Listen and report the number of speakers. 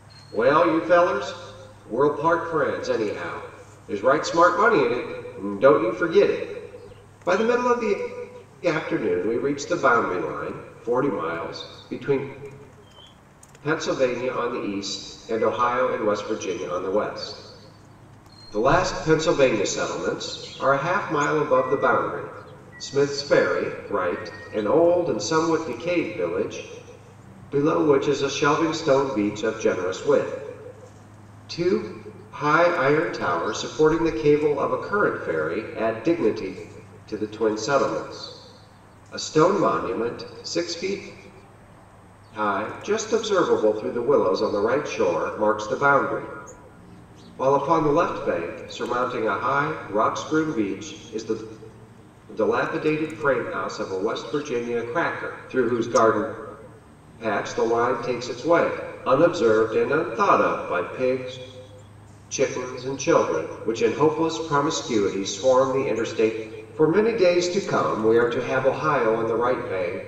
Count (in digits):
1